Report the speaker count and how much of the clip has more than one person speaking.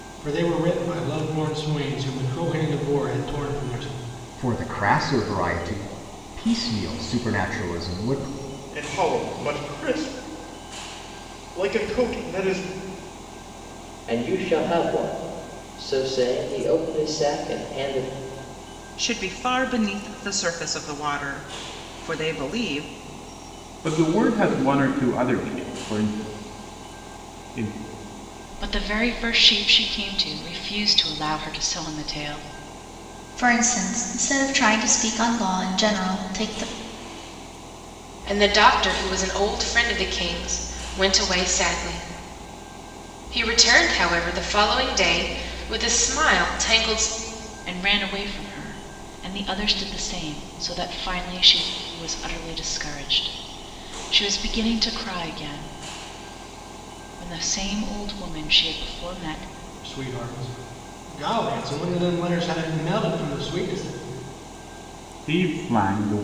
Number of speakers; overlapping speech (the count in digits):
9, no overlap